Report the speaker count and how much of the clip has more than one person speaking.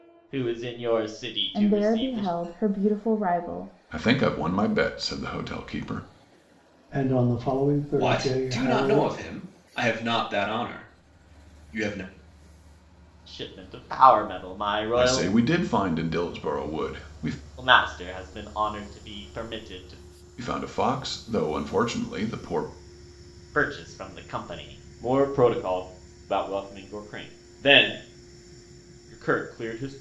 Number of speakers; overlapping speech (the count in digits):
5, about 8%